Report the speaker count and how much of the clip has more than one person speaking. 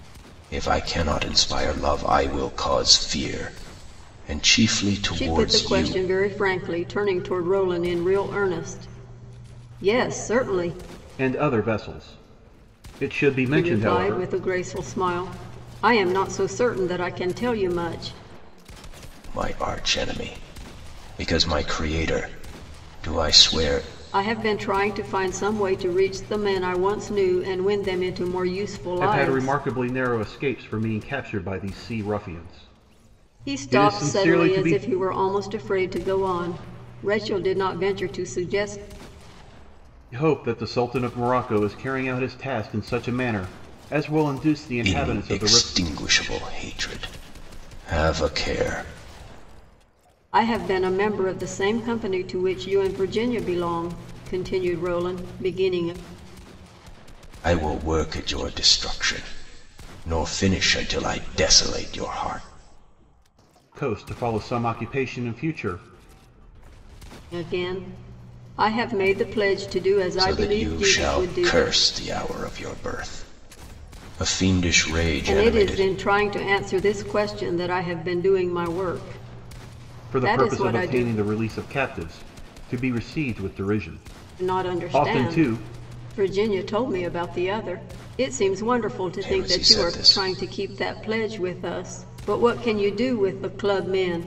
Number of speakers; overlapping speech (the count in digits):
3, about 11%